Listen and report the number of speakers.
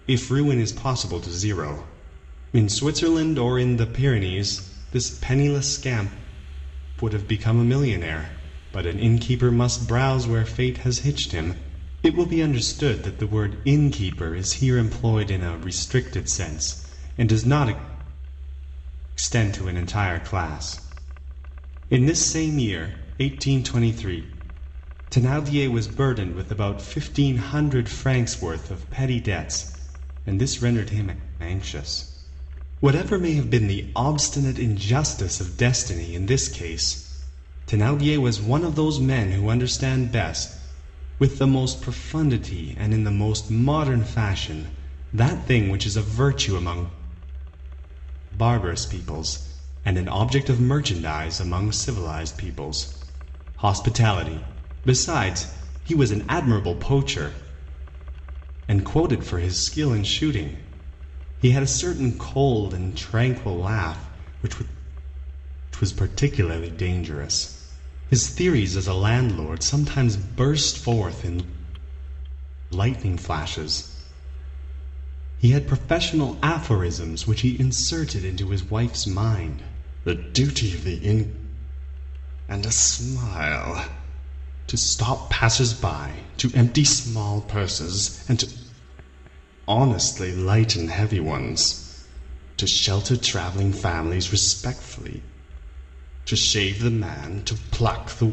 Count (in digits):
1